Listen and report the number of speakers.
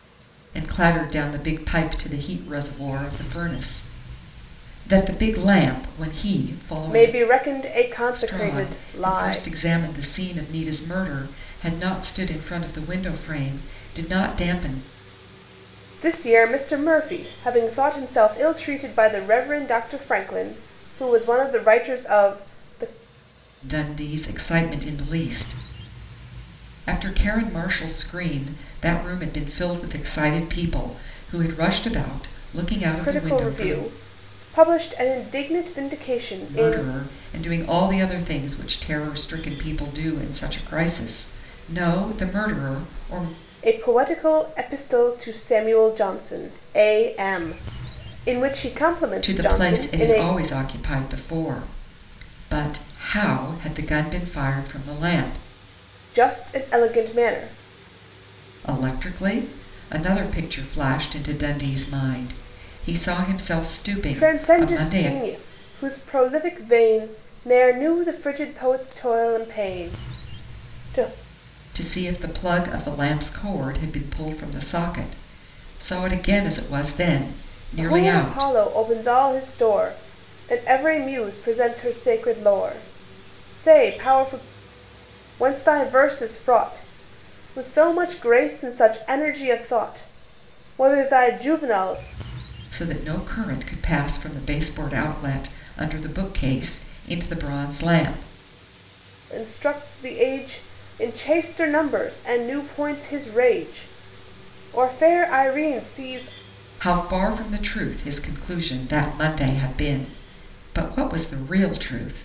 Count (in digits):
2